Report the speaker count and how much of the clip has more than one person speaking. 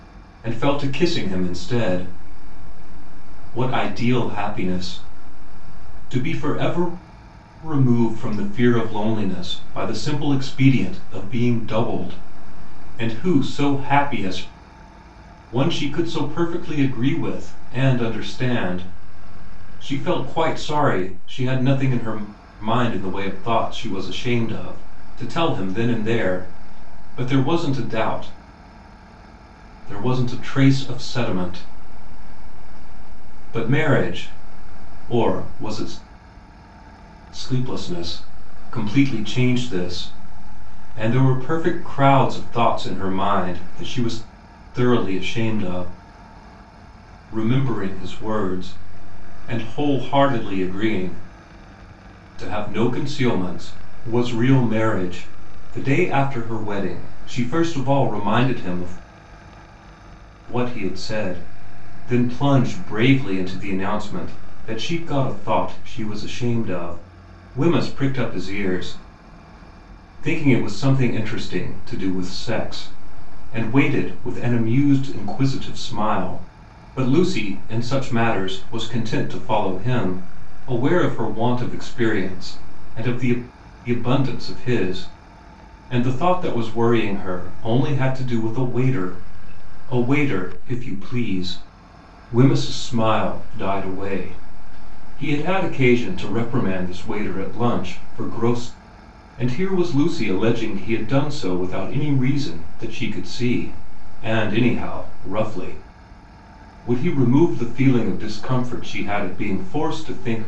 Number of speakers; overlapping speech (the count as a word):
one, no overlap